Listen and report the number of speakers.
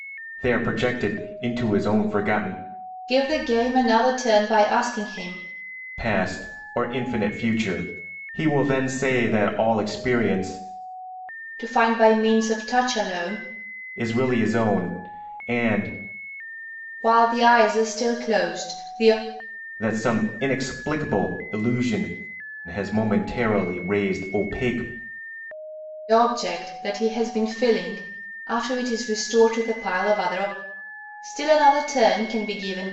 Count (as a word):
two